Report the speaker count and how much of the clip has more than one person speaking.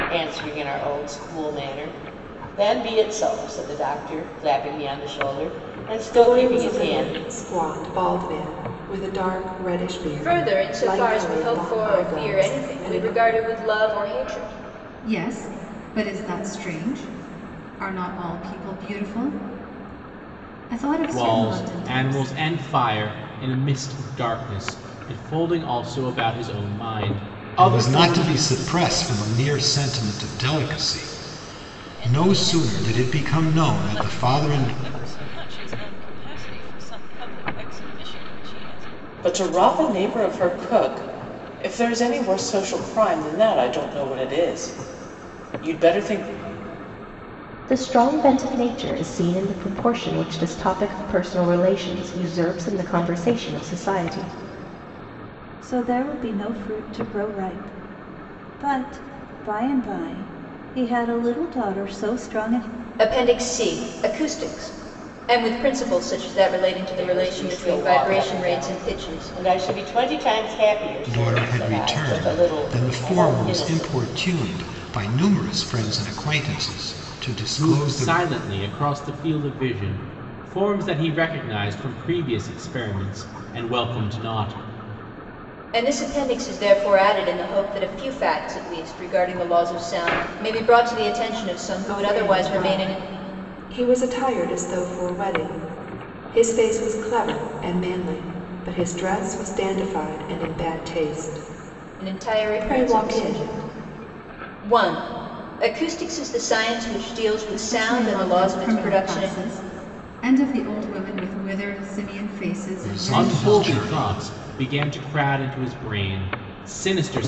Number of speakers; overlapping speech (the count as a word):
ten, about 18%